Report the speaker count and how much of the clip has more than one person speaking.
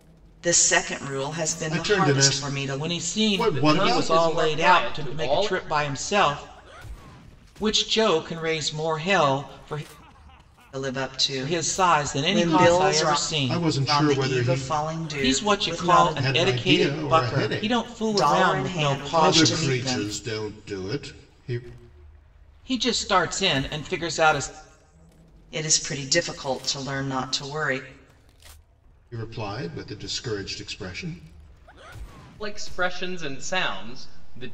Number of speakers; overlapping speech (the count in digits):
4, about 33%